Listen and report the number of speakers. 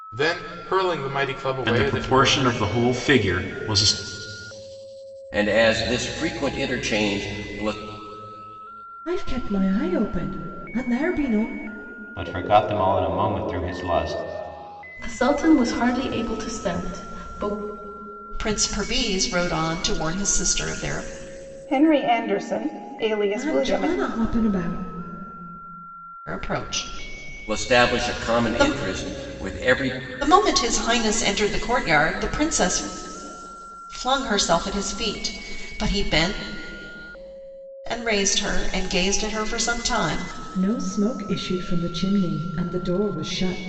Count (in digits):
8